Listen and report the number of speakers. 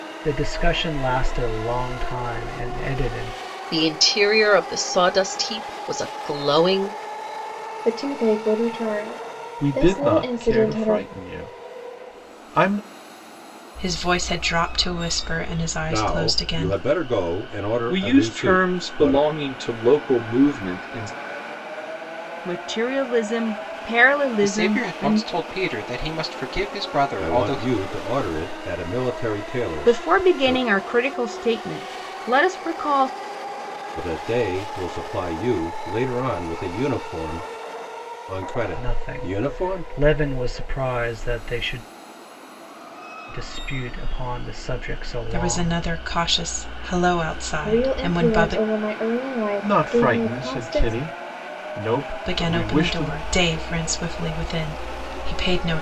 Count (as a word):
nine